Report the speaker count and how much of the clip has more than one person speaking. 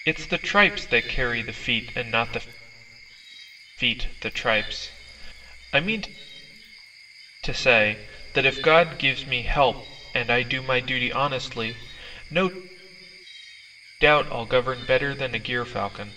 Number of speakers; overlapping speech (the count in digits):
1, no overlap